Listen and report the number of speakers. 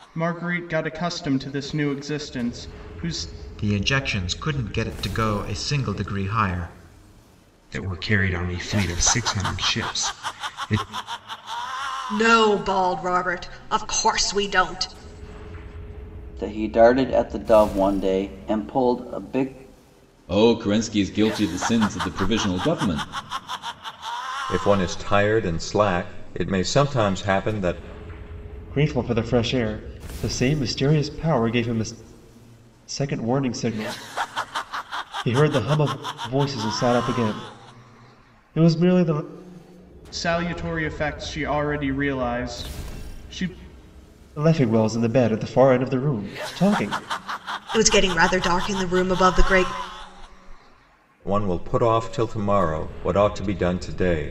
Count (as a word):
eight